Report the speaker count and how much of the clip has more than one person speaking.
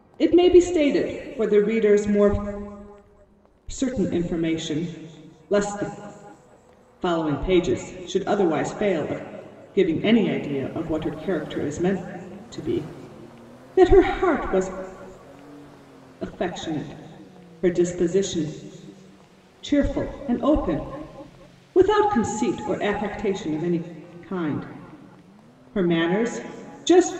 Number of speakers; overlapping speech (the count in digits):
1, no overlap